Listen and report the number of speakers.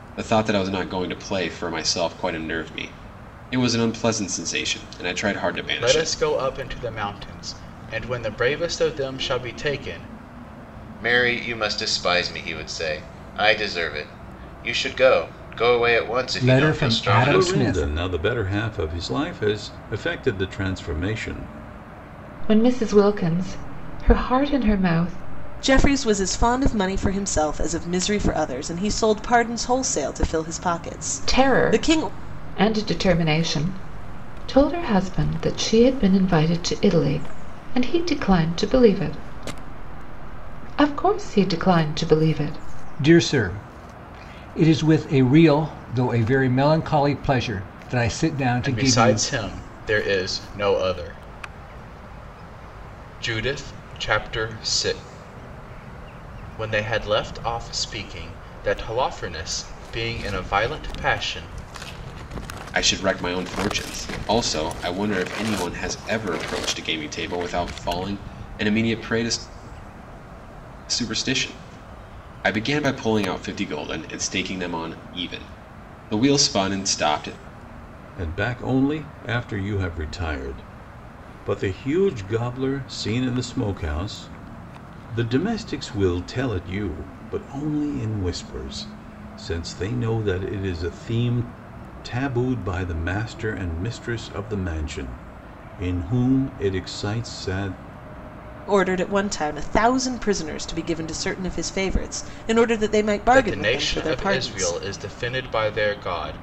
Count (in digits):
7